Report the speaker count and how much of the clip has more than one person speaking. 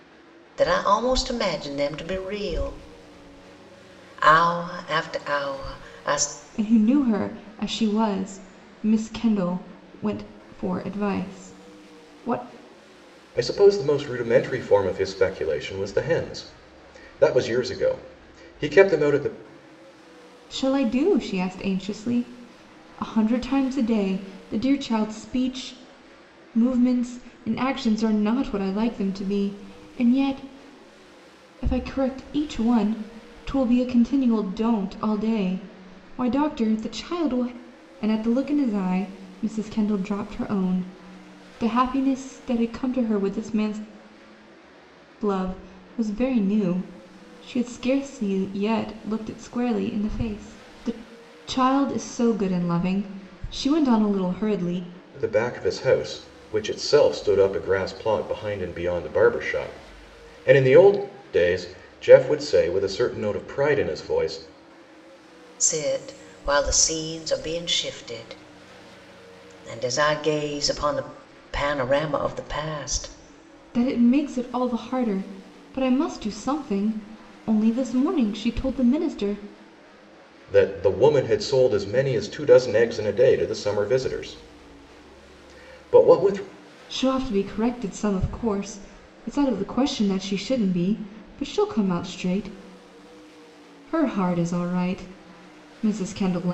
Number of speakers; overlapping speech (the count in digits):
3, no overlap